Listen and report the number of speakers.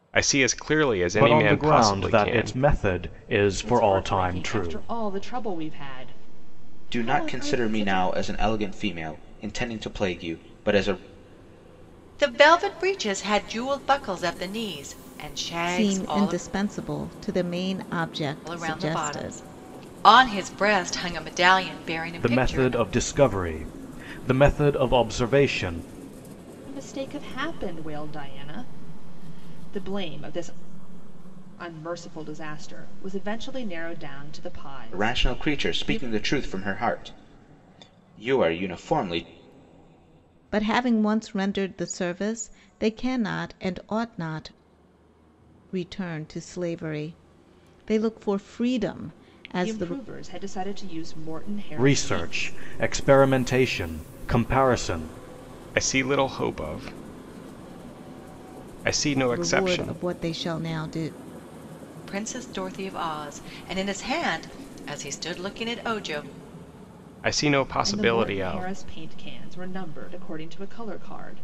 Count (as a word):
six